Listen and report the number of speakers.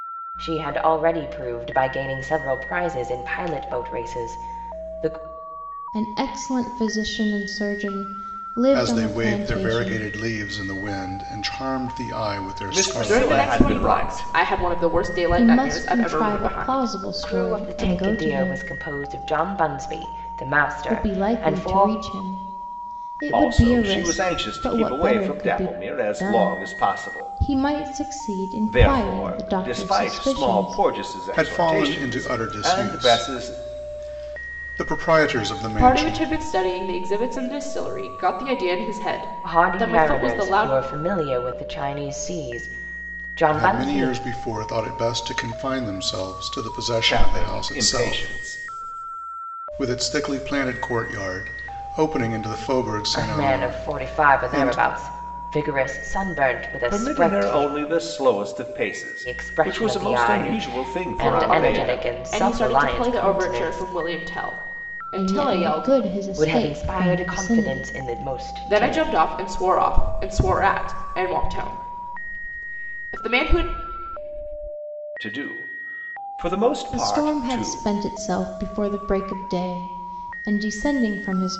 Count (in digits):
5